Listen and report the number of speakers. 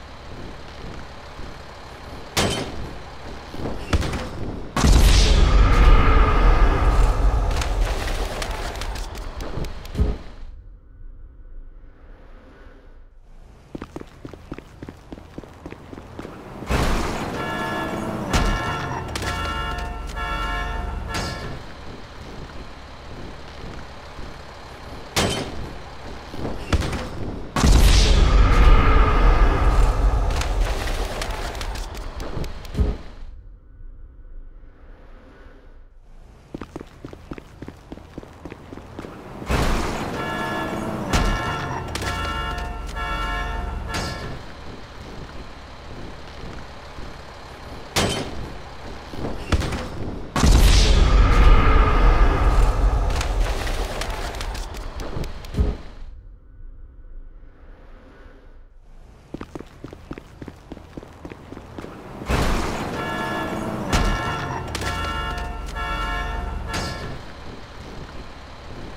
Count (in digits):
0